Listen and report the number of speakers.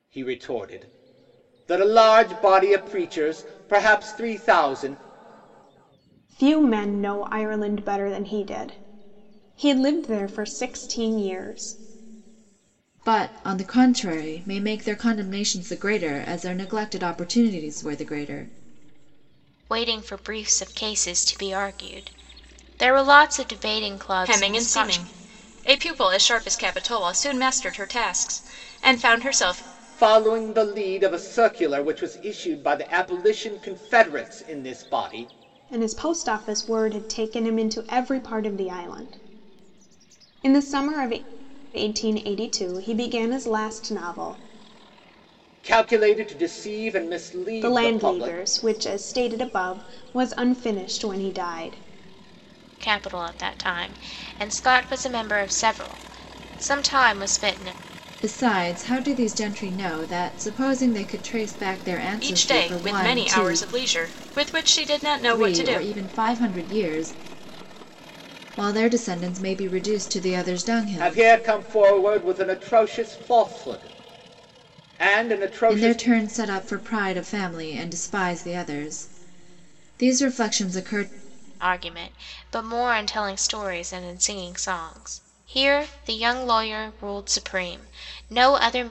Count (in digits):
5